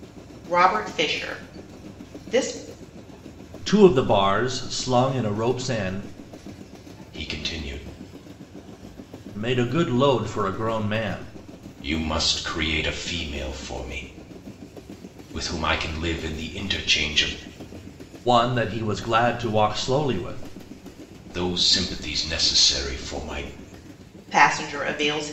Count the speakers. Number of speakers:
3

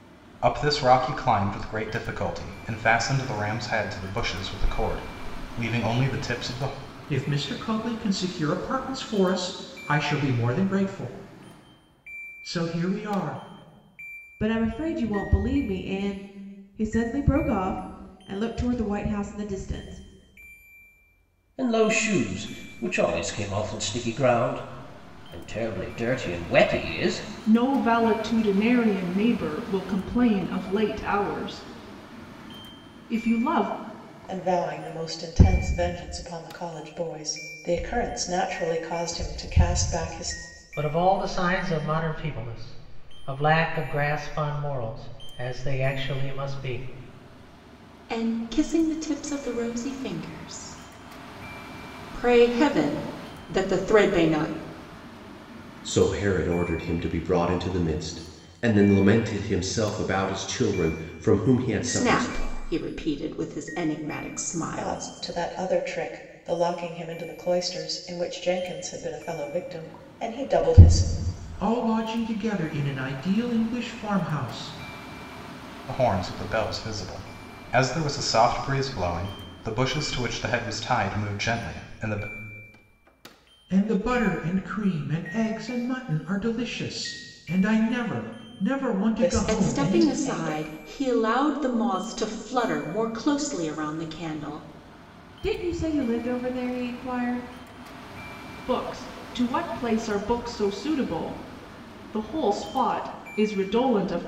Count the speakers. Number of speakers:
9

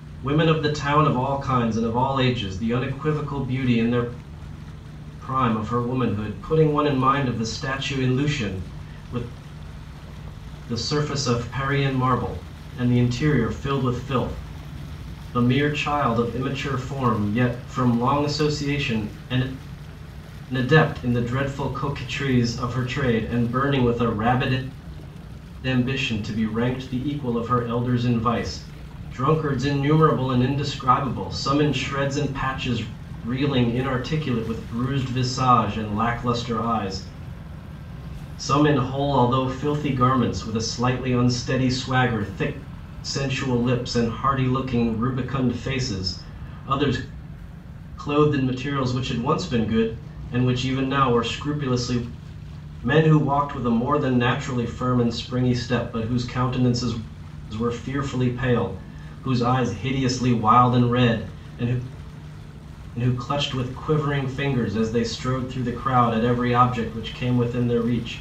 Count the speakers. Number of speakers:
1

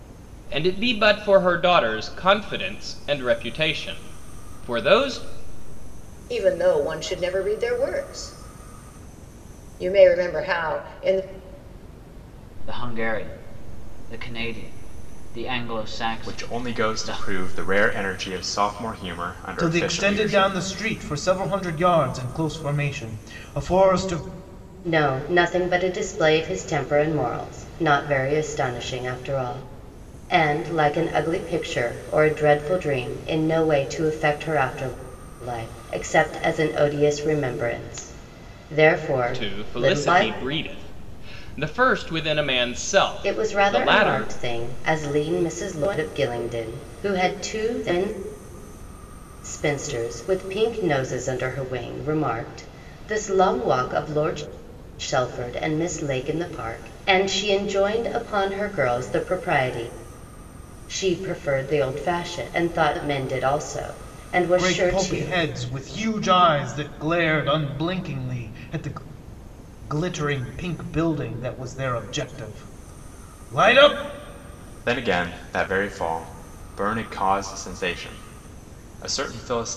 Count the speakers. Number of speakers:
6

